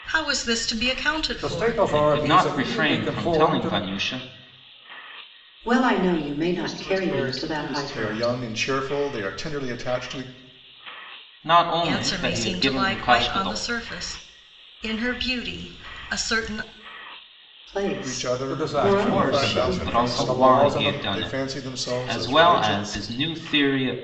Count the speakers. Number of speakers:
6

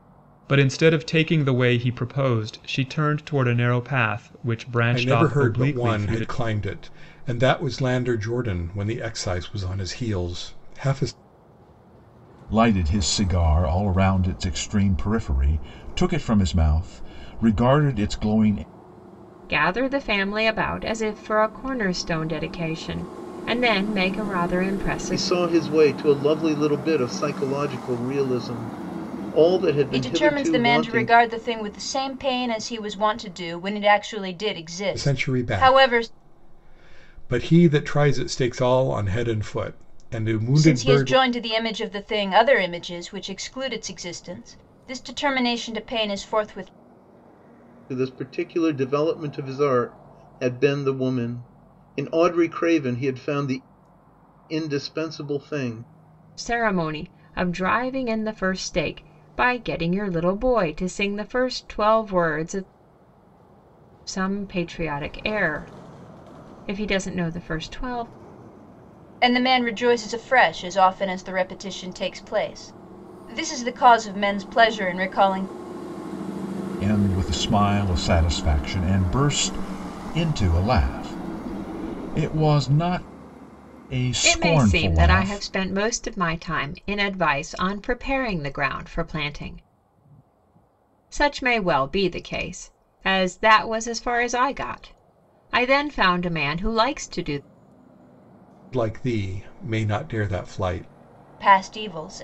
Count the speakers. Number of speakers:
6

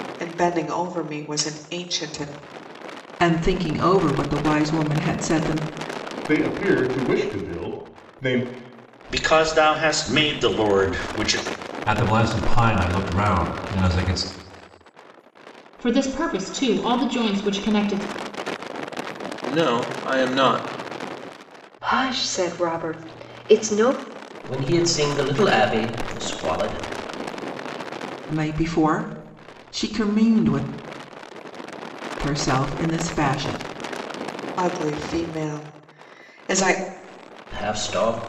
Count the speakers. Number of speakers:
9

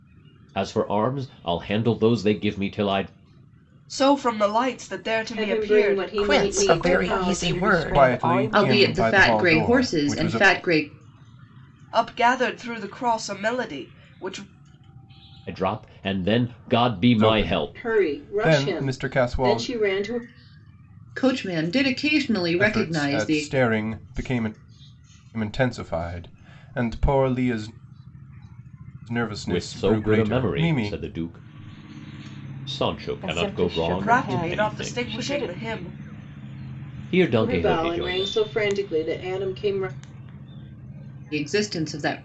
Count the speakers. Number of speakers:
7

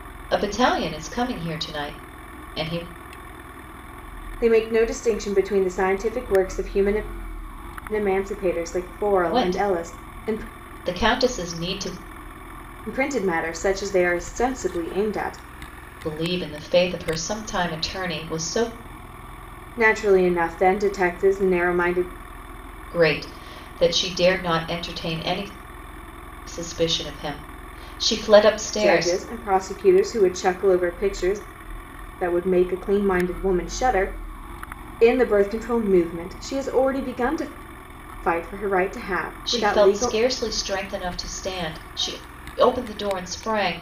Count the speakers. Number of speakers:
2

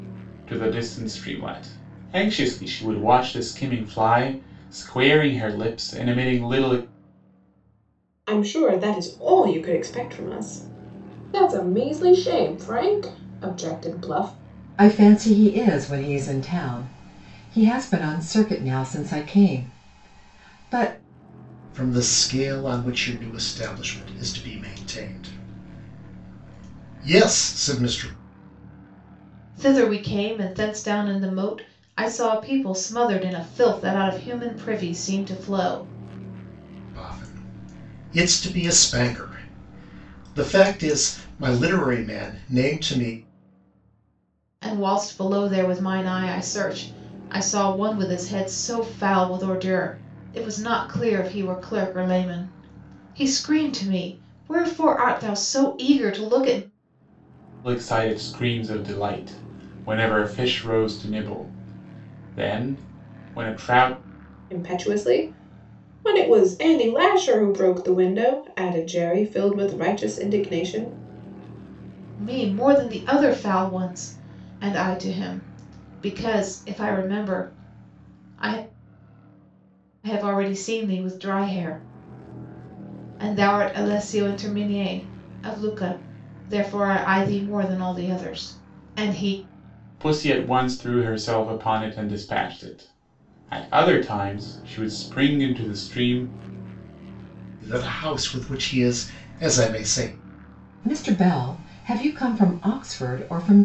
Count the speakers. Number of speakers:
5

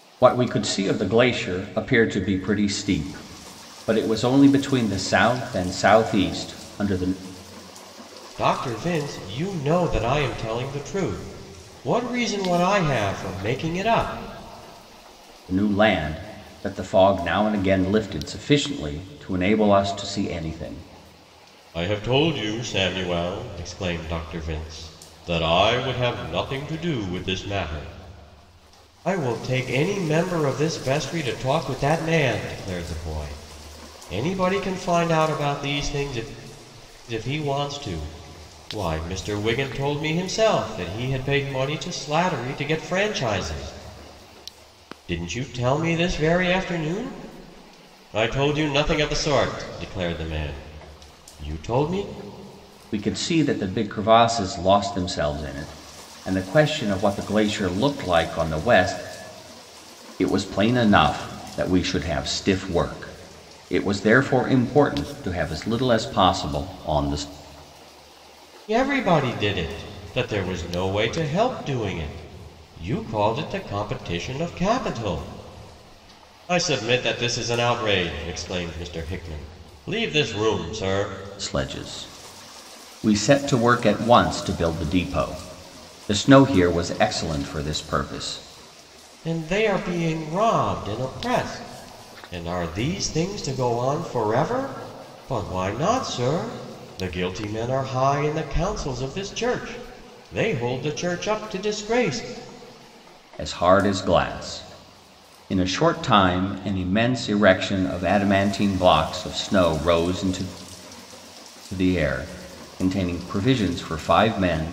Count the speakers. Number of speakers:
2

